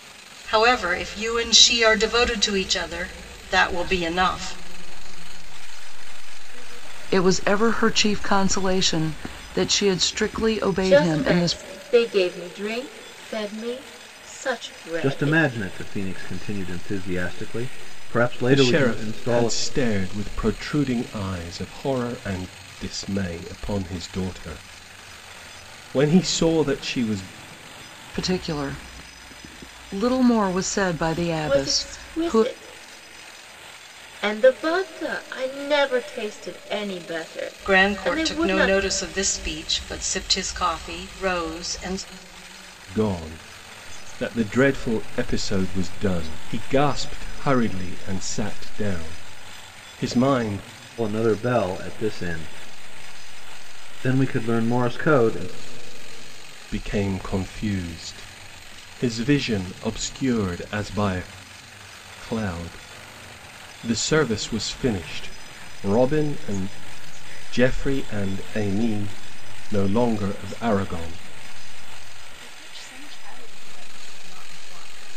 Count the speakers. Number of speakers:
six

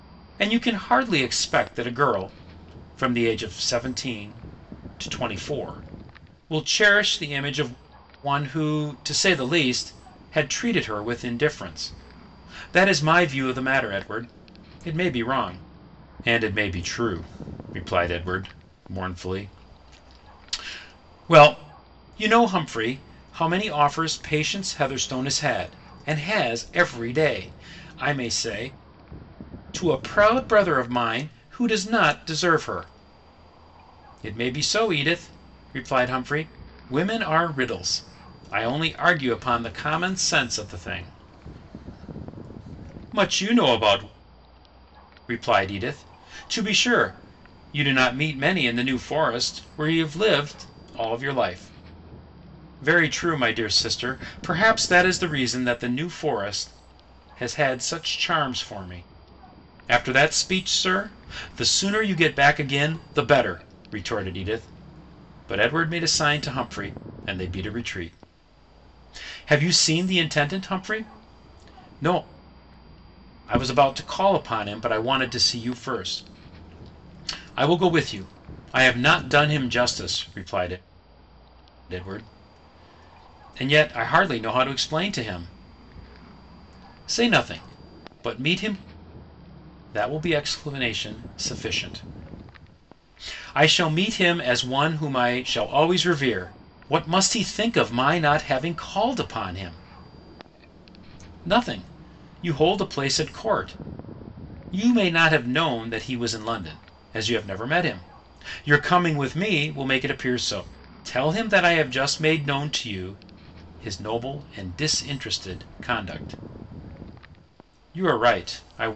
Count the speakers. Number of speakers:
one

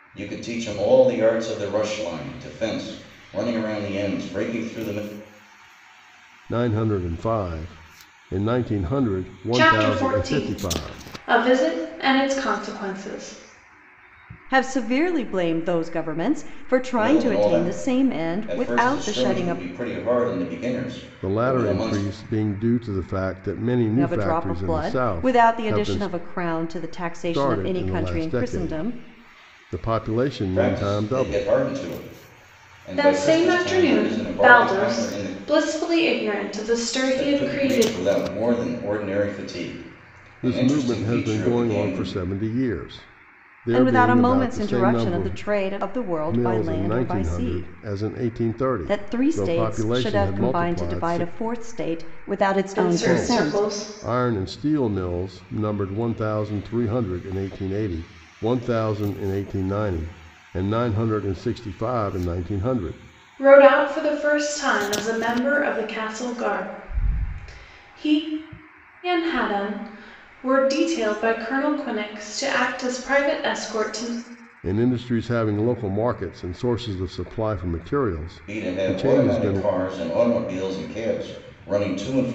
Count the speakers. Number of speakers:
four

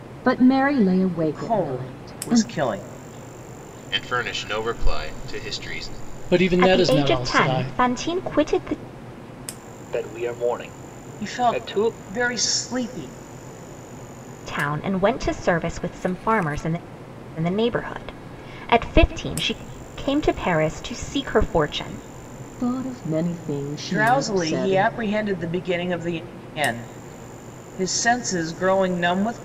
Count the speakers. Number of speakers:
six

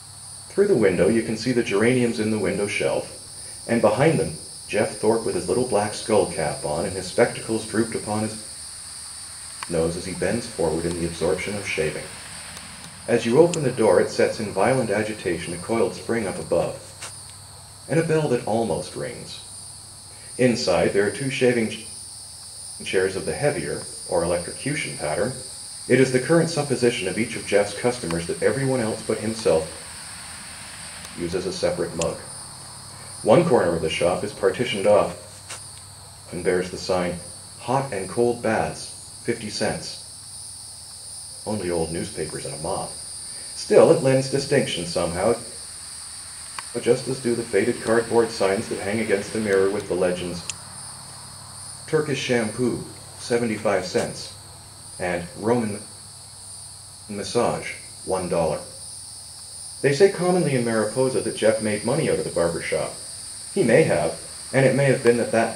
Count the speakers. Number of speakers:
one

